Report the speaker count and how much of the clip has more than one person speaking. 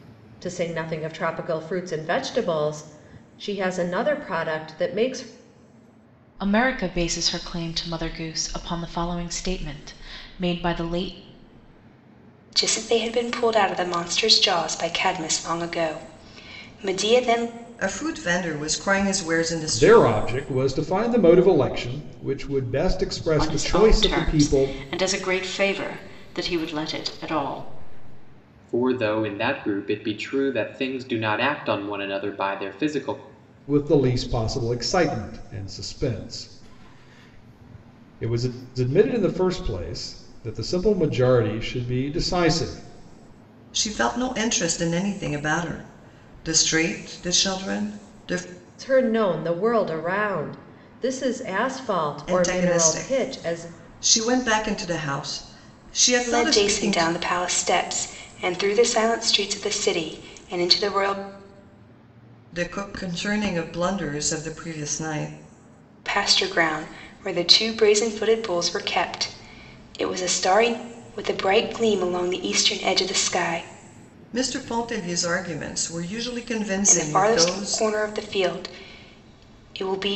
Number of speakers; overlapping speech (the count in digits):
7, about 7%